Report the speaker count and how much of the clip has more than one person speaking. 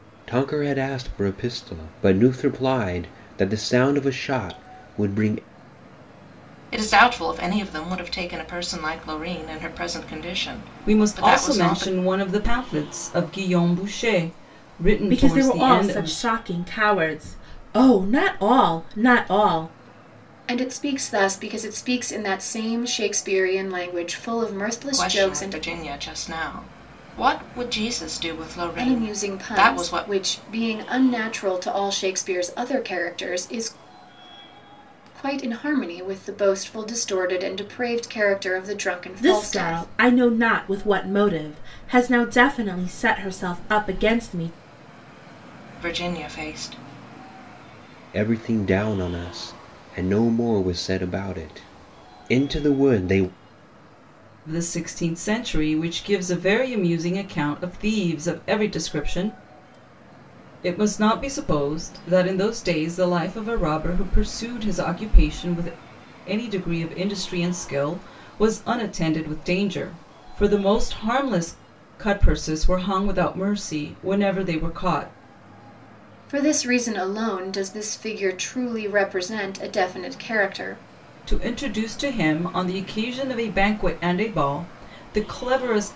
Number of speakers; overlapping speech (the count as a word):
five, about 6%